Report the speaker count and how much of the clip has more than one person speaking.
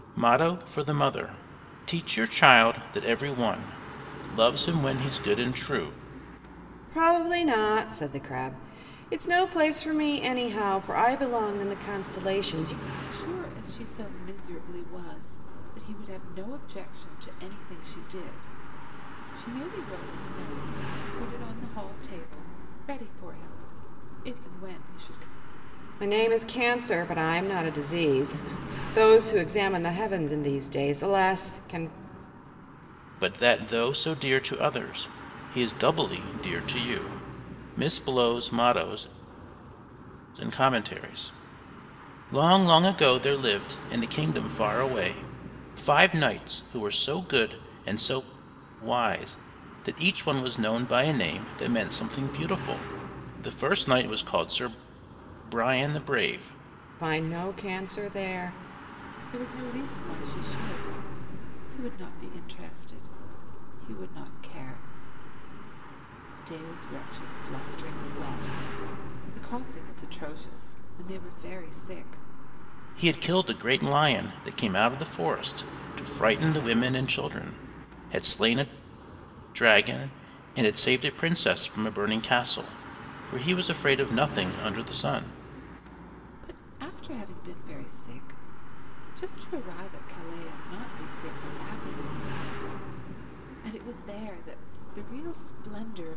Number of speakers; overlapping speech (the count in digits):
3, no overlap